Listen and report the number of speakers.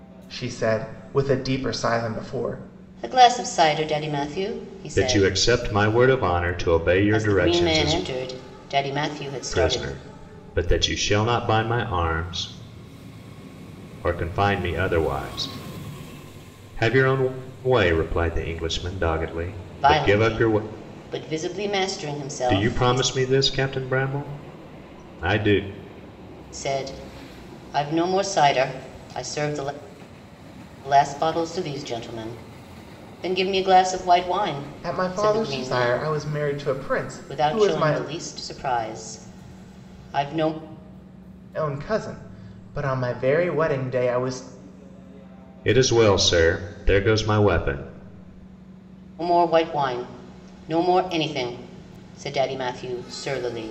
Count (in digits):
3